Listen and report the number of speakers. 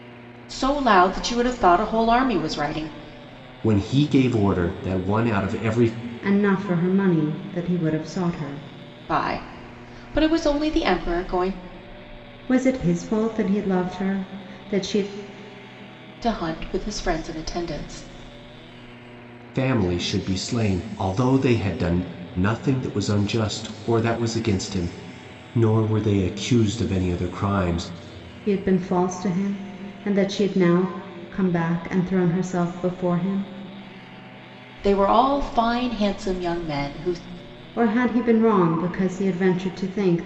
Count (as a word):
three